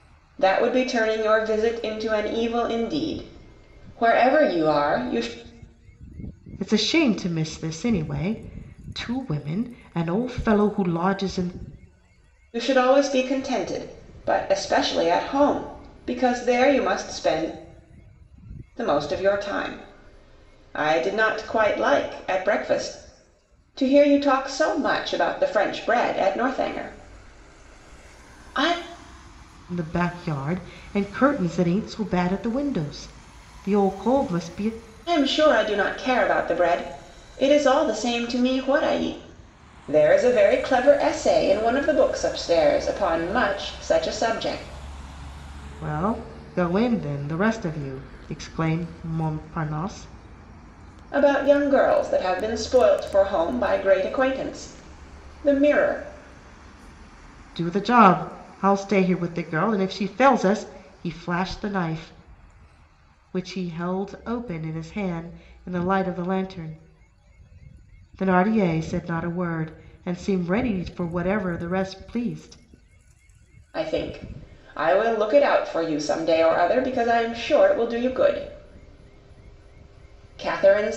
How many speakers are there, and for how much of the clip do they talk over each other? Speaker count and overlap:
2, no overlap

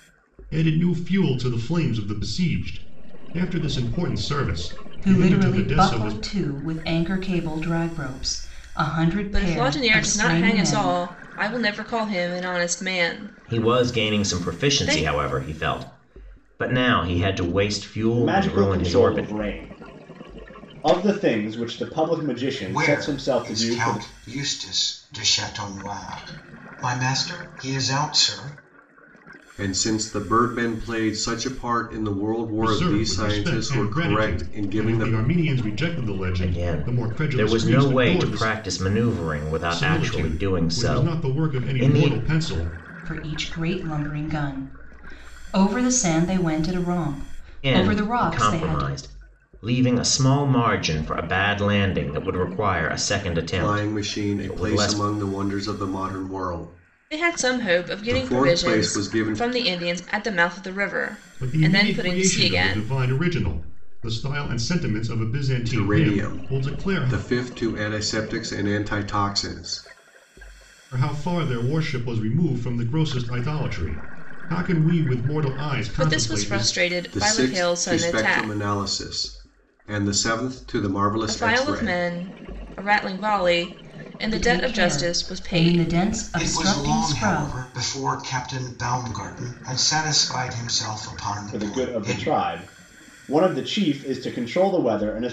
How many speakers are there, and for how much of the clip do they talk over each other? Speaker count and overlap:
7, about 31%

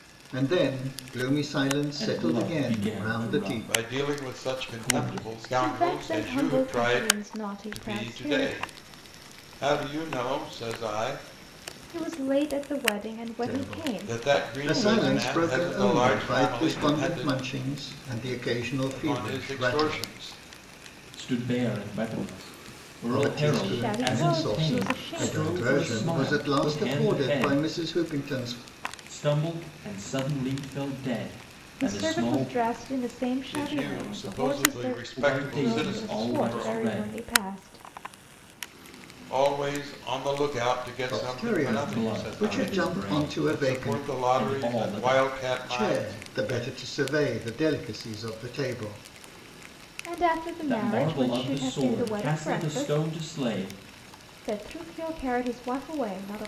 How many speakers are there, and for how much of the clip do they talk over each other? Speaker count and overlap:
4, about 50%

